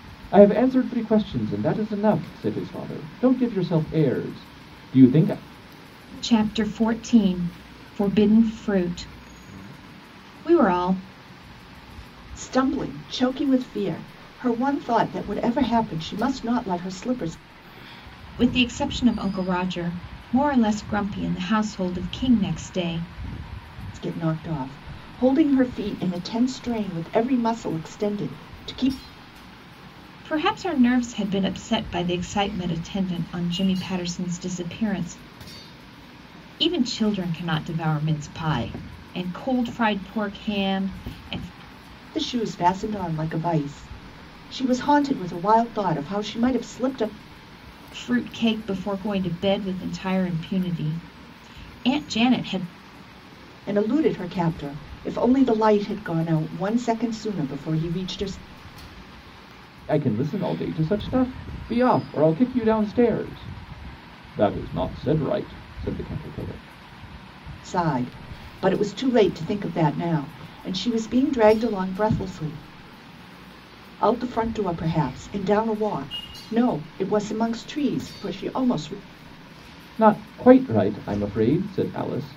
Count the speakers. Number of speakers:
three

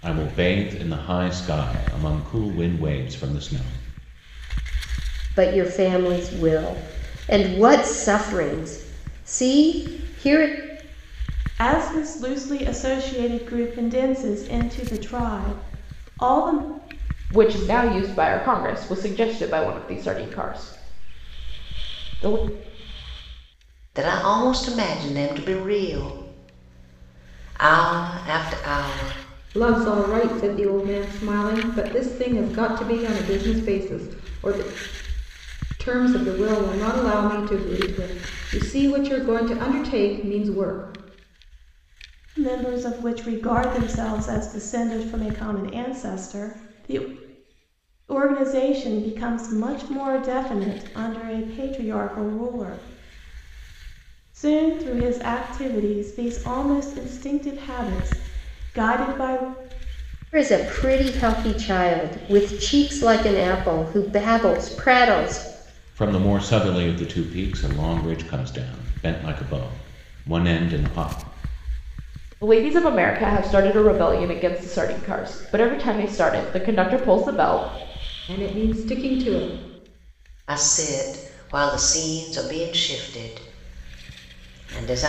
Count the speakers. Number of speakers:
six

